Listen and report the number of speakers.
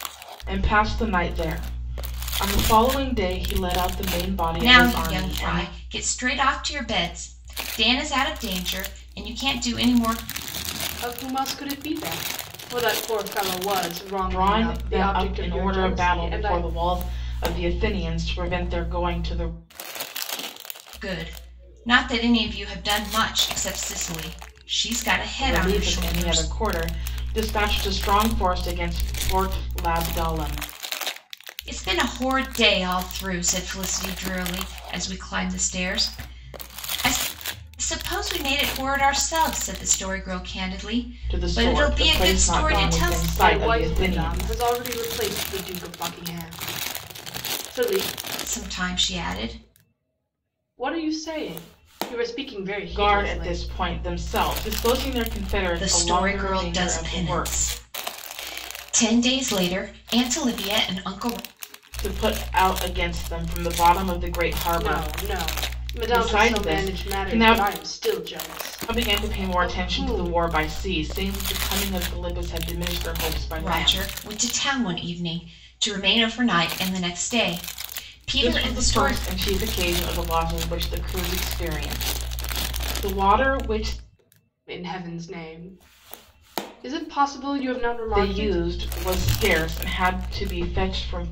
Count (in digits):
3